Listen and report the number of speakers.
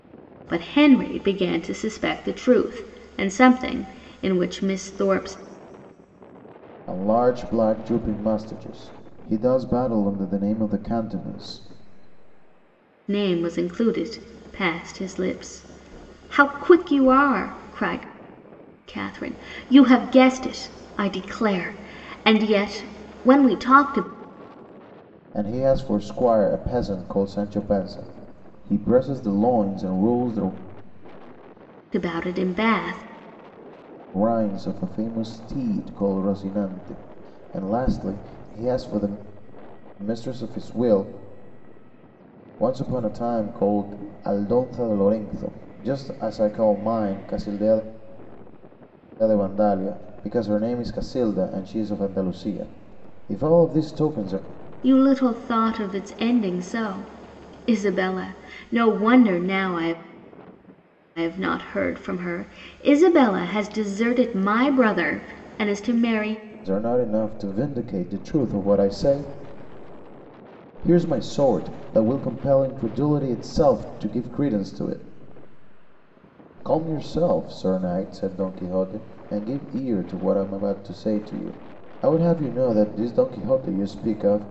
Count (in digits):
2